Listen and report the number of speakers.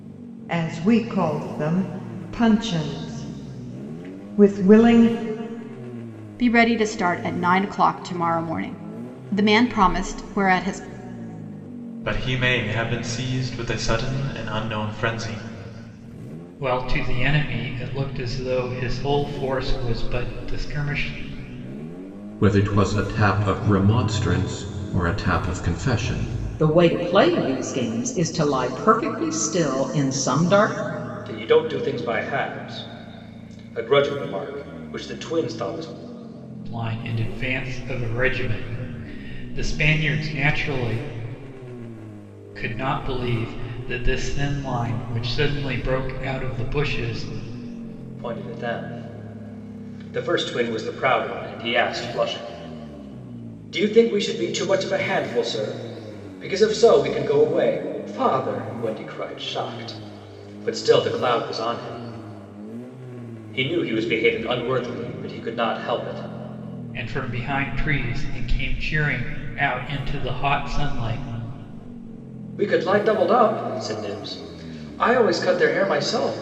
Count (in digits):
7